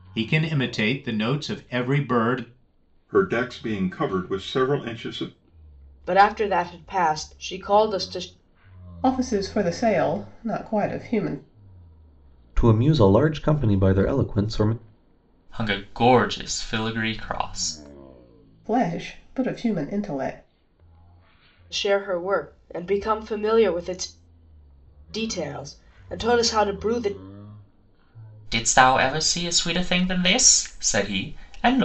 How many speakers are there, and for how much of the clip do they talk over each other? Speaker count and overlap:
six, no overlap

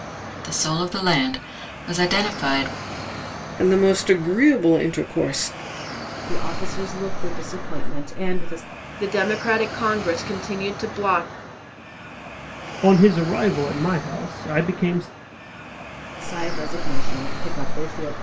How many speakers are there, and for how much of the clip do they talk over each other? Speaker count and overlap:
five, no overlap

